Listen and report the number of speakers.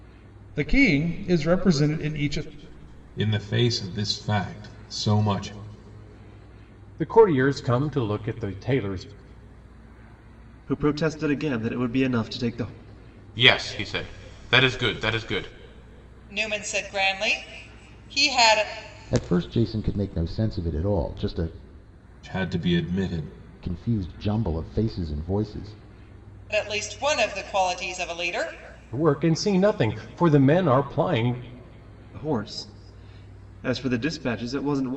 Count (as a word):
seven